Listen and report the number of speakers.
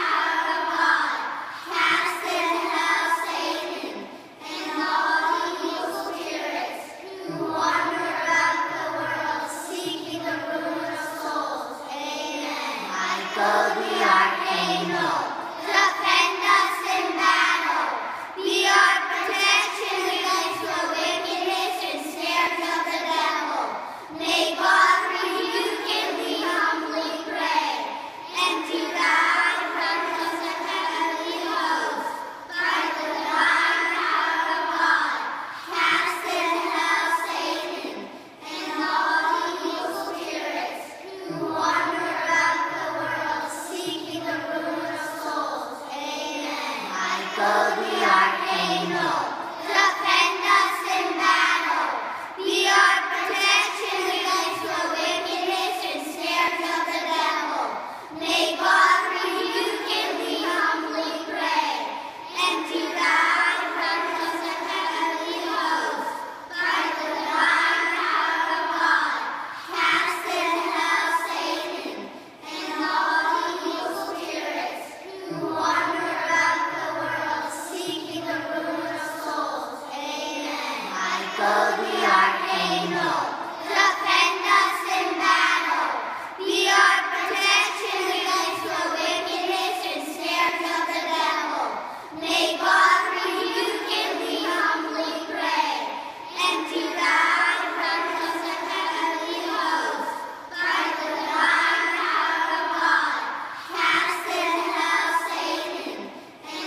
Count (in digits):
0